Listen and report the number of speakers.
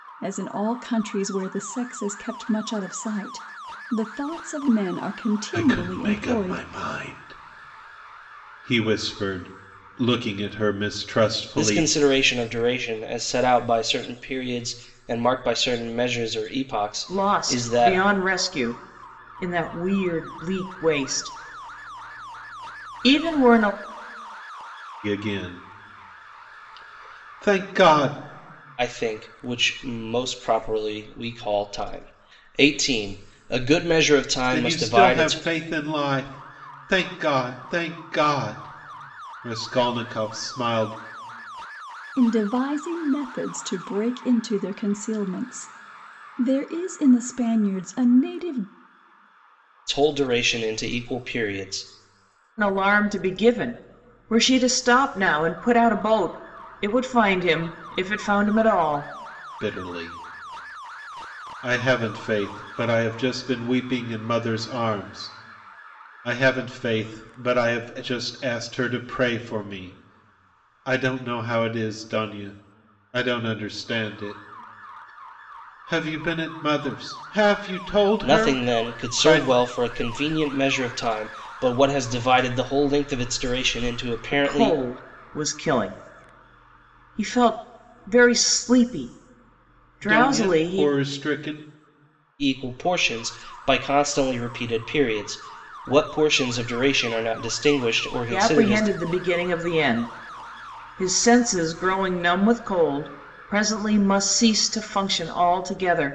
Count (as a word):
four